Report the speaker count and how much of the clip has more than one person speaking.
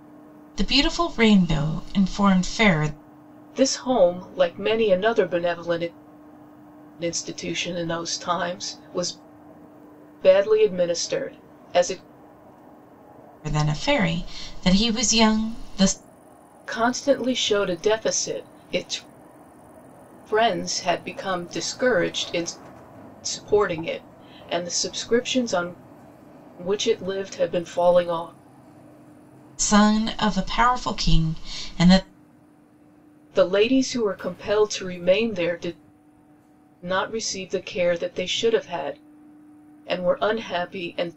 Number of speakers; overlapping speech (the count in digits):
2, no overlap